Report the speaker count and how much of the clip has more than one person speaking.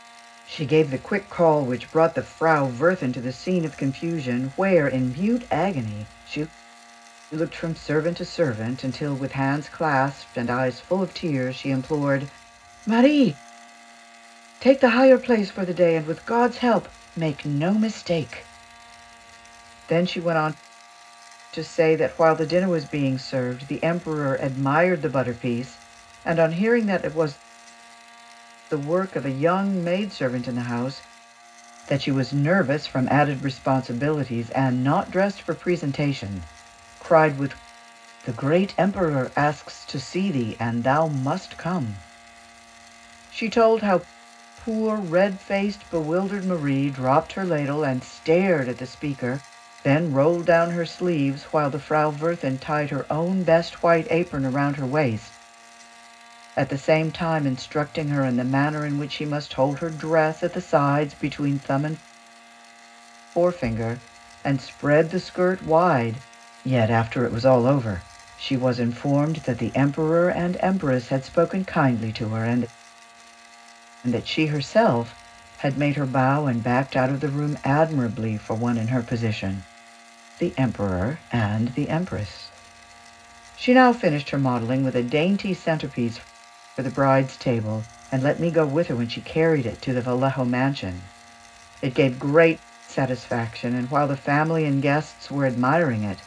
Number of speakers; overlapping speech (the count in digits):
1, no overlap